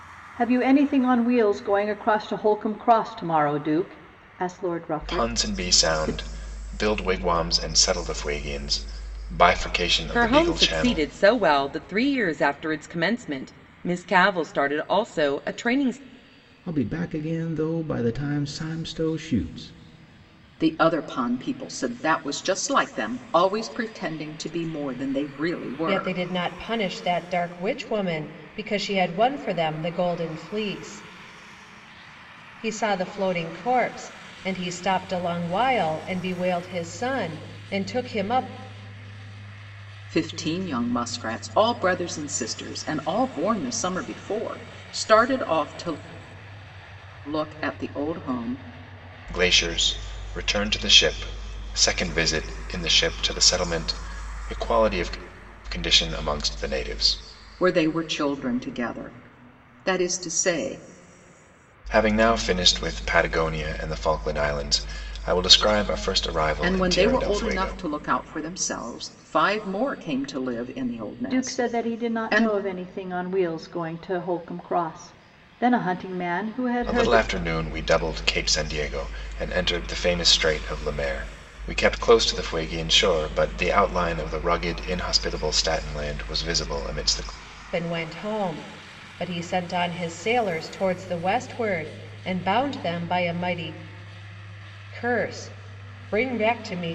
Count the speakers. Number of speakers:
6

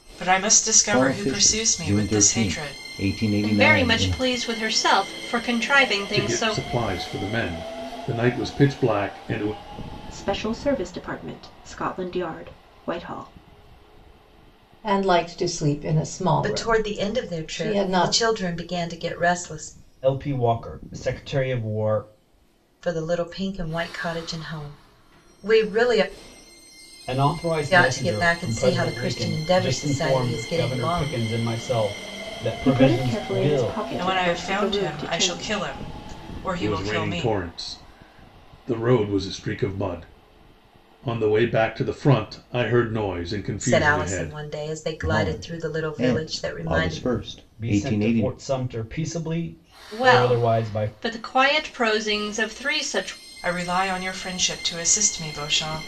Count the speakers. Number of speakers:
8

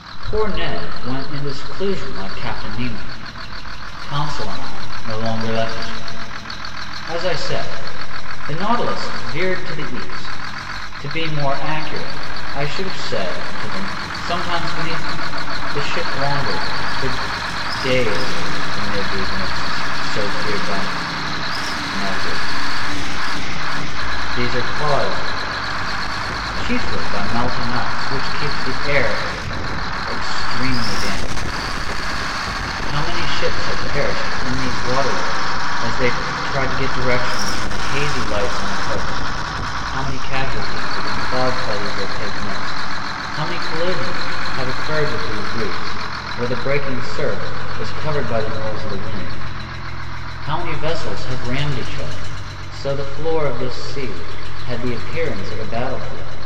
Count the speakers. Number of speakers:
1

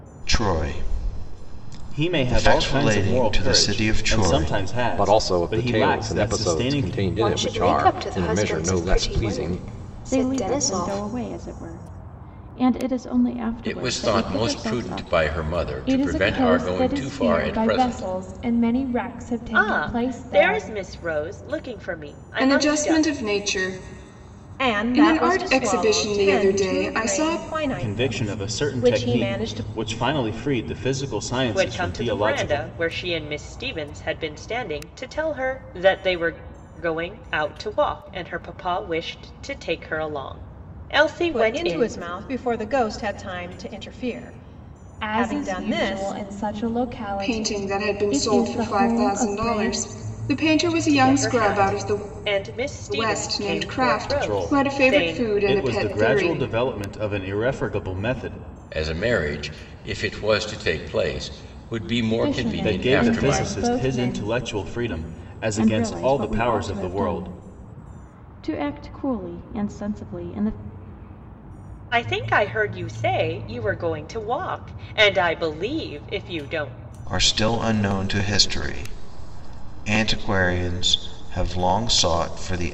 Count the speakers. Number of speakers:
10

